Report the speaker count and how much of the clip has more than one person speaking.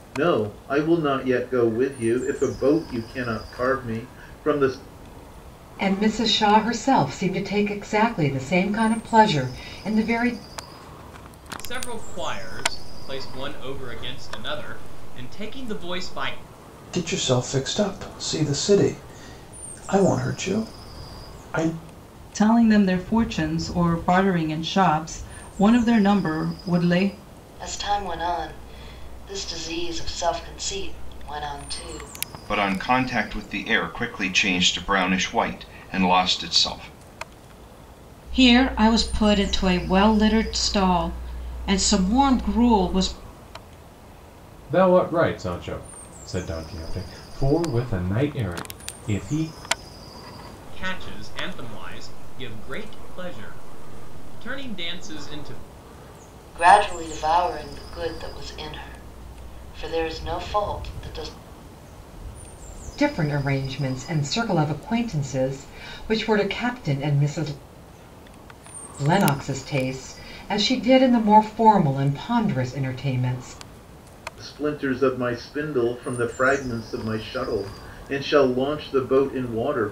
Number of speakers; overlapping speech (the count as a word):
nine, no overlap